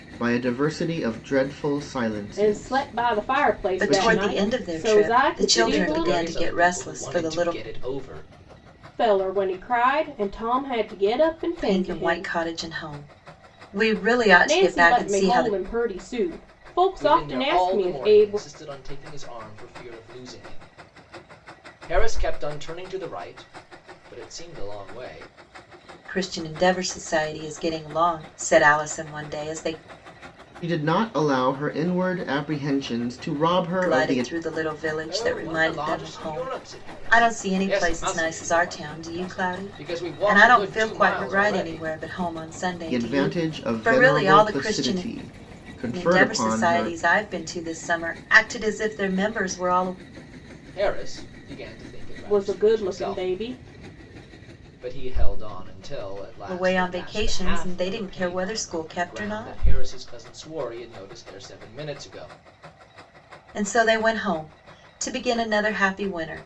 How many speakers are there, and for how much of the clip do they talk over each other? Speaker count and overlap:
four, about 34%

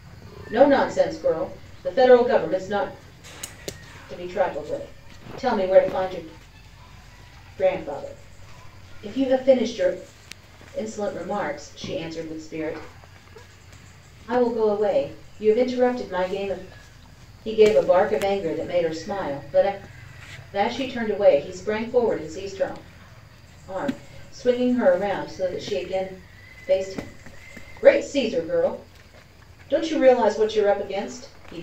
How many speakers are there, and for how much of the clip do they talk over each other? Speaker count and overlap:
one, no overlap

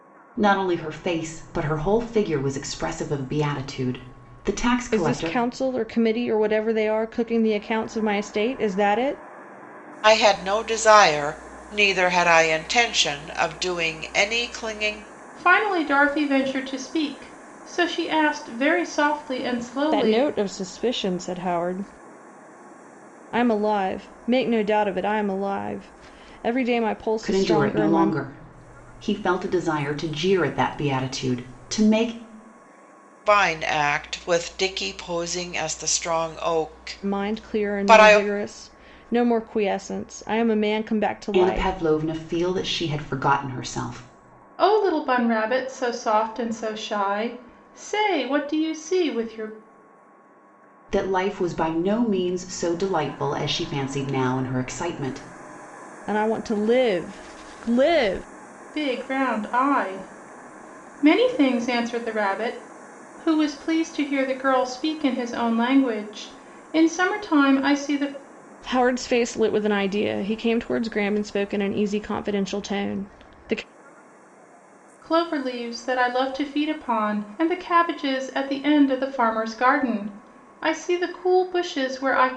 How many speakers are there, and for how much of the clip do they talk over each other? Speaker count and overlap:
four, about 4%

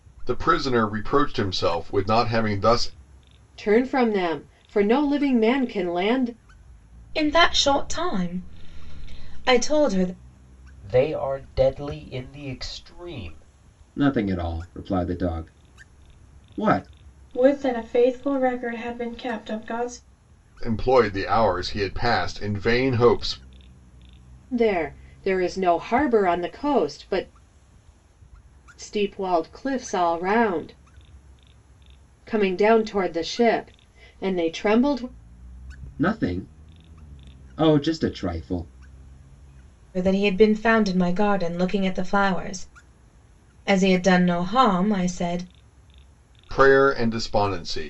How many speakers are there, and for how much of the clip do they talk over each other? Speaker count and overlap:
six, no overlap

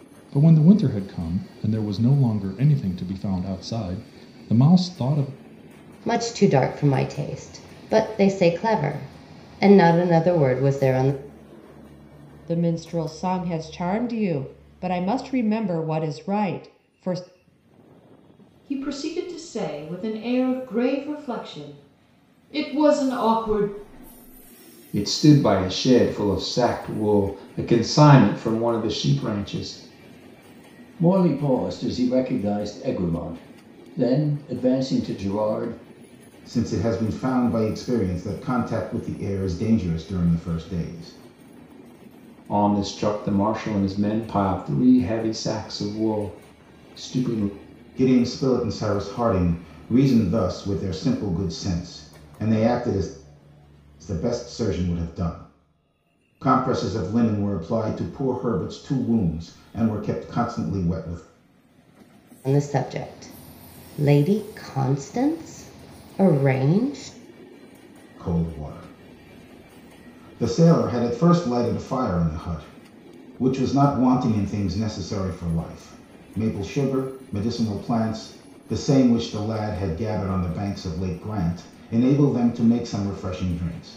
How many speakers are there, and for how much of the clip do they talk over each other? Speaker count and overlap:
seven, no overlap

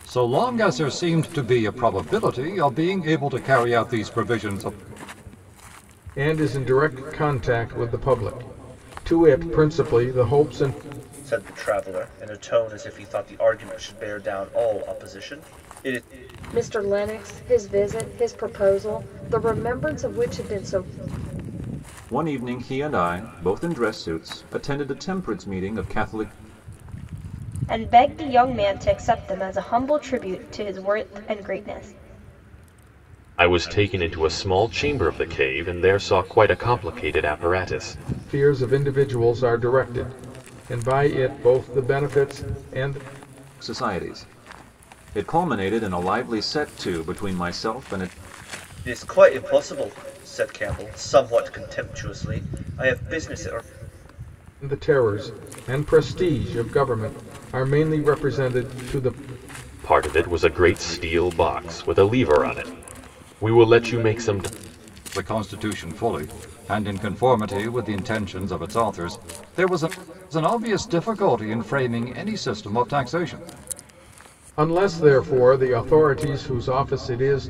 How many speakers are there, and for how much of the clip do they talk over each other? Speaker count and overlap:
seven, no overlap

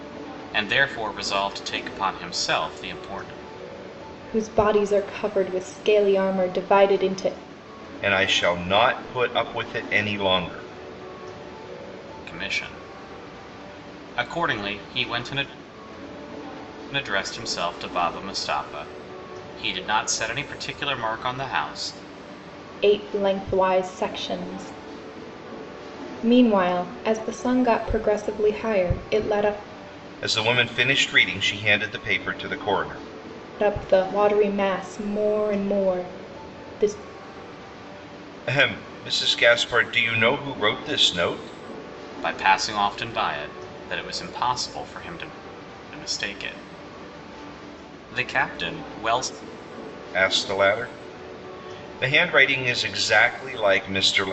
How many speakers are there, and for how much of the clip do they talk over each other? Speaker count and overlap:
three, no overlap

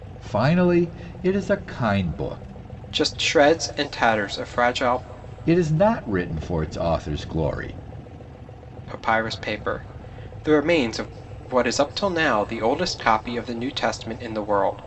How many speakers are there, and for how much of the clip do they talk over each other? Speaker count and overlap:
two, no overlap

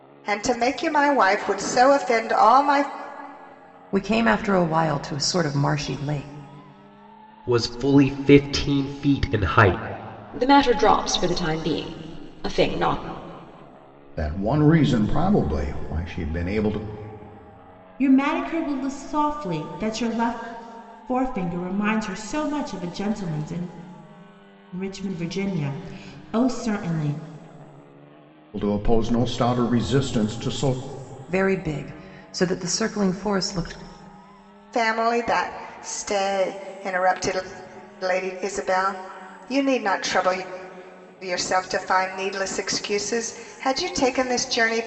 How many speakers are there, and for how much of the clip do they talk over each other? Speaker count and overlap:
six, no overlap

